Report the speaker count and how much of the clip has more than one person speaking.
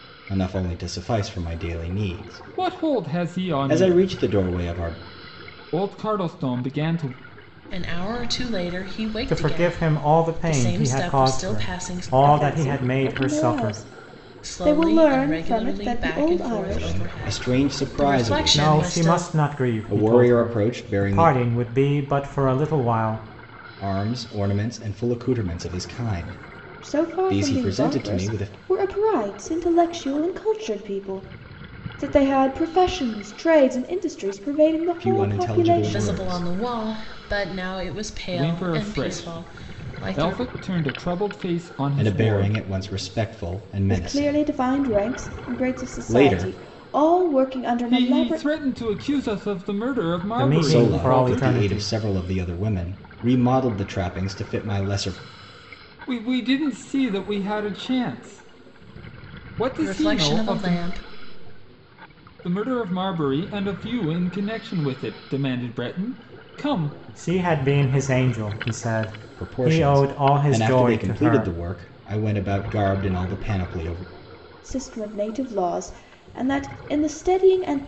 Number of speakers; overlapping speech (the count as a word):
five, about 36%